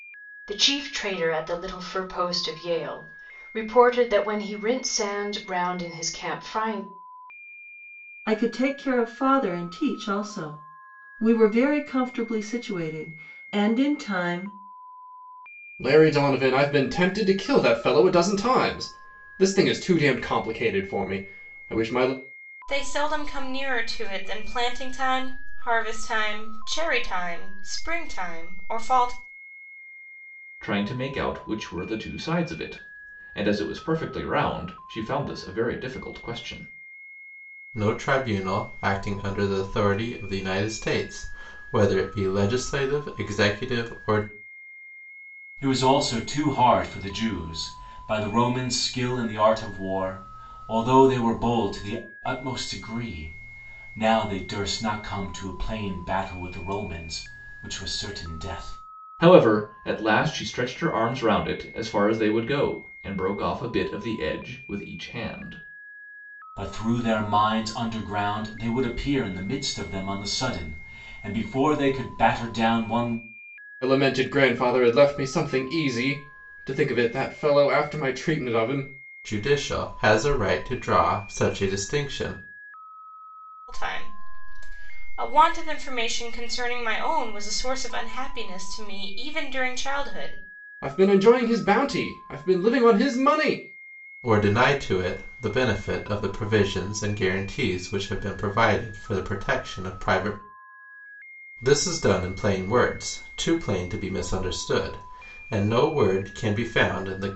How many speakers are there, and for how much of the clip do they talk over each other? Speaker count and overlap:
7, no overlap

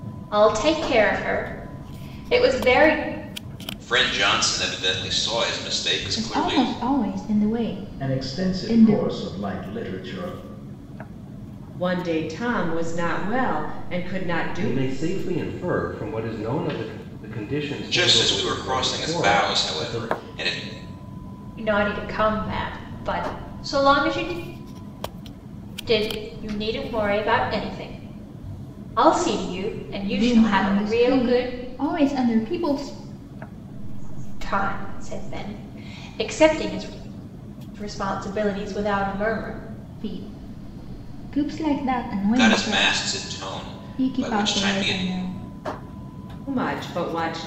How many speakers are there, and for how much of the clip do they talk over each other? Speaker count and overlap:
7, about 23%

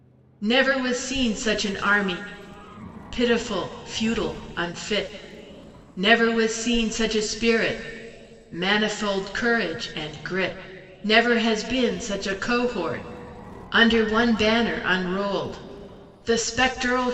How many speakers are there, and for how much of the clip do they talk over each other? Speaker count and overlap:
1, no overlap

